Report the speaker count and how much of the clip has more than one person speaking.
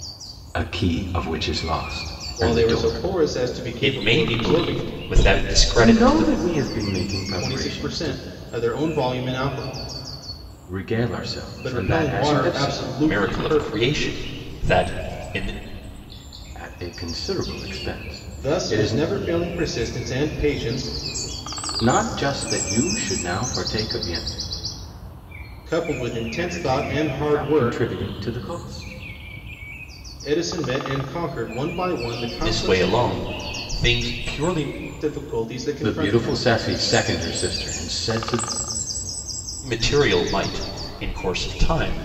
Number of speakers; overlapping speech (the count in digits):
3, about 21%